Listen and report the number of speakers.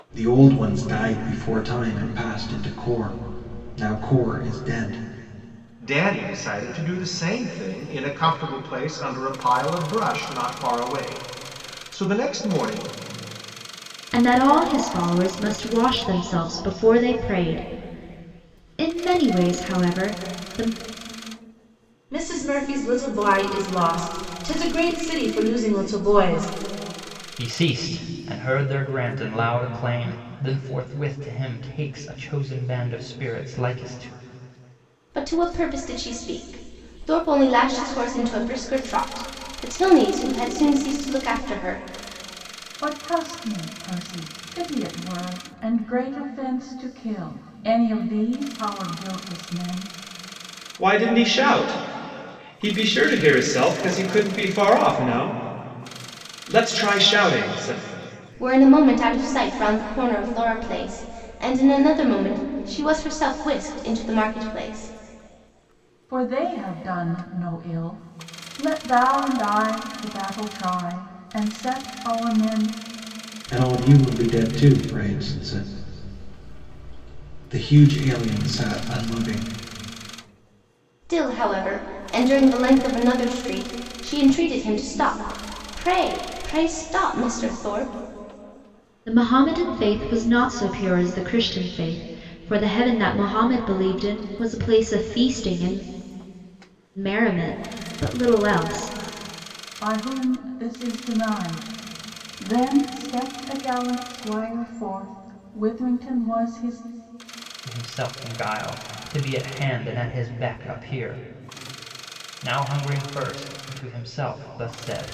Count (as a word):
eight